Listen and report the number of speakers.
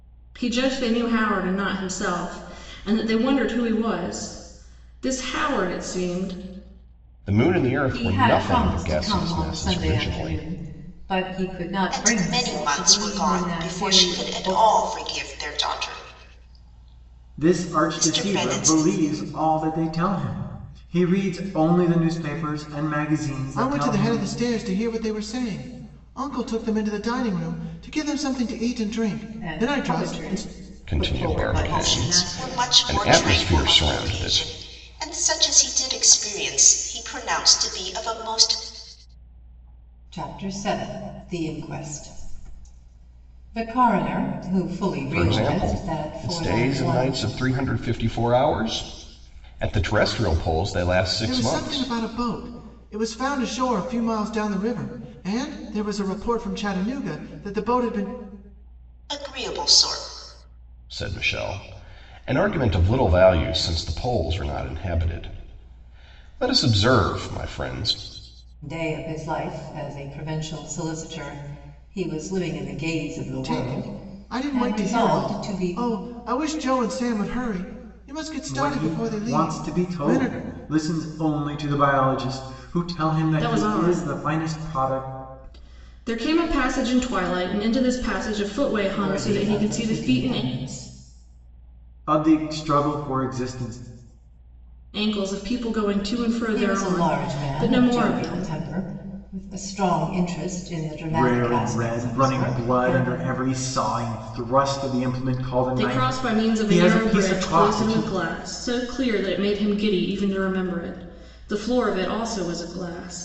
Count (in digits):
6